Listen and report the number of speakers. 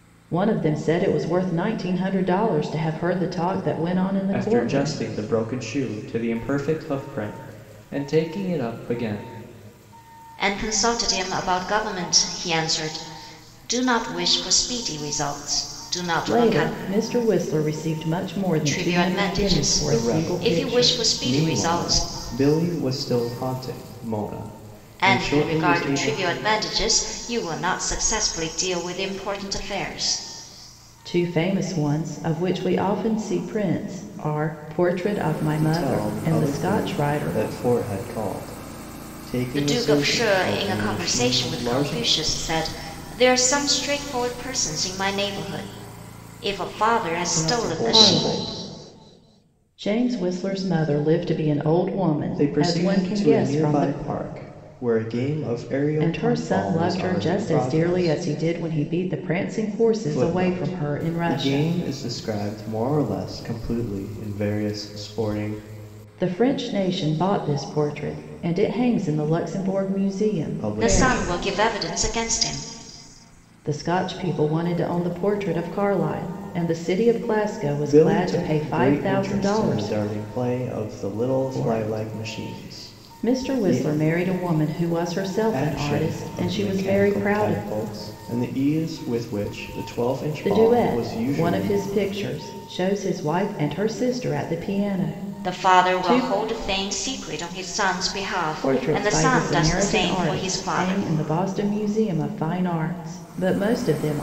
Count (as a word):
three